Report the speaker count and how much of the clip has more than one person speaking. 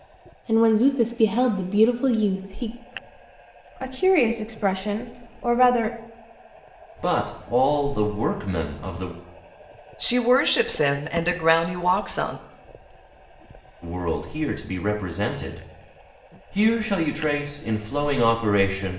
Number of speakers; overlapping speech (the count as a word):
four, no overlap